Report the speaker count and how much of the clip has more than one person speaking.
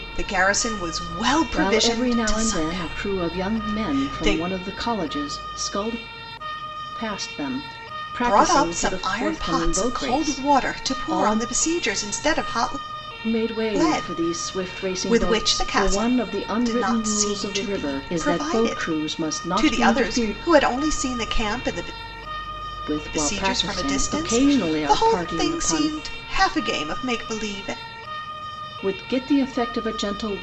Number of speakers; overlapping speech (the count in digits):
2, about 49%